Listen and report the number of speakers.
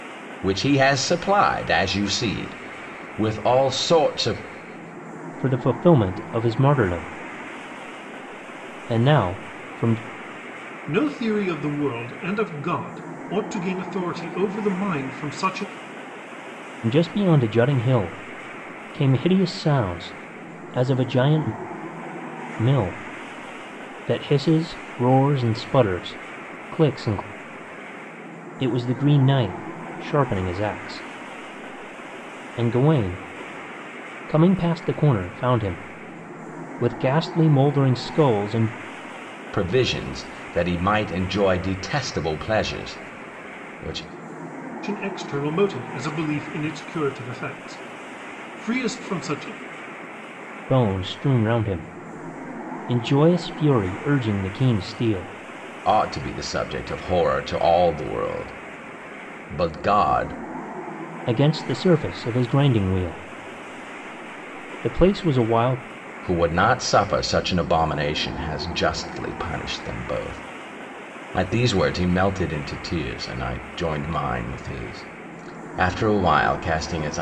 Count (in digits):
3